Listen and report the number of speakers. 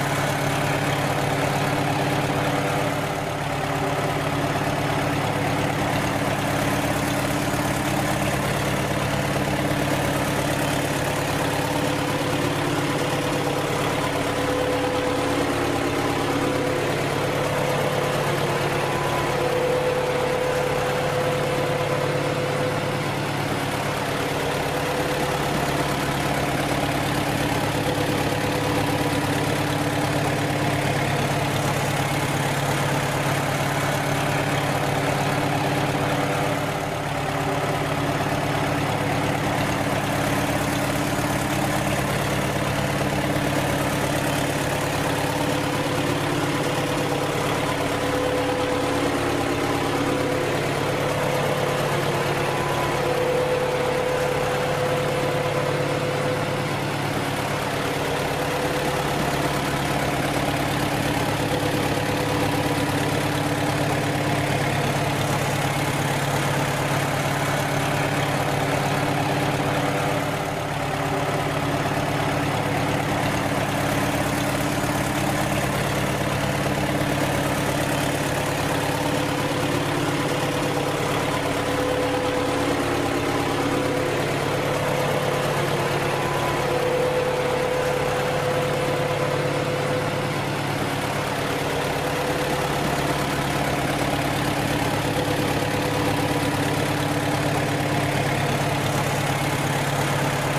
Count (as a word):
zero